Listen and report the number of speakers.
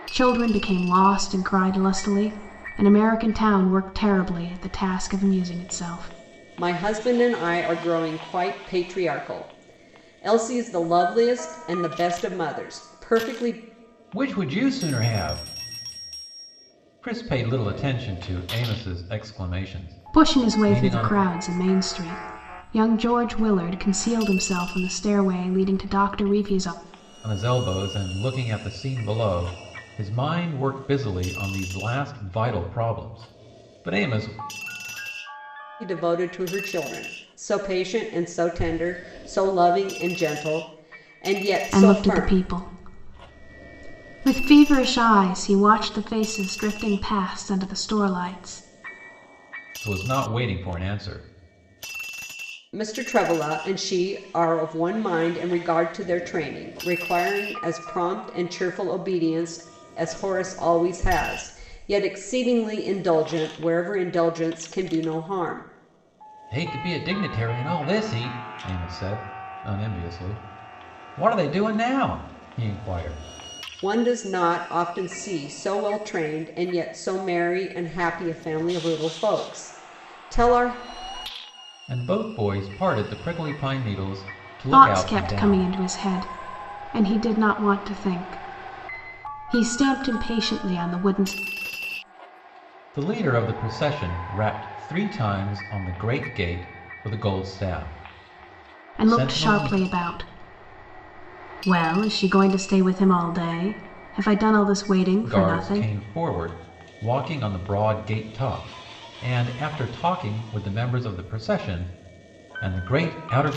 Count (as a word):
three